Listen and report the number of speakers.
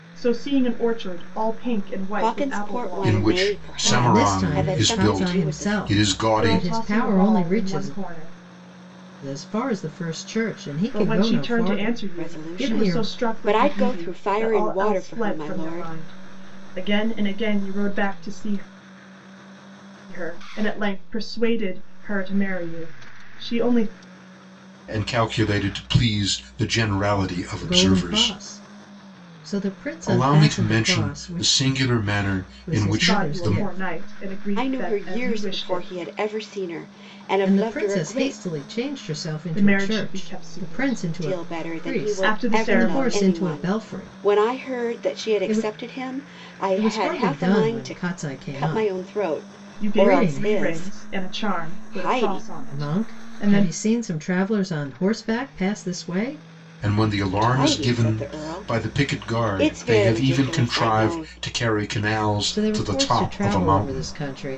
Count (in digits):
4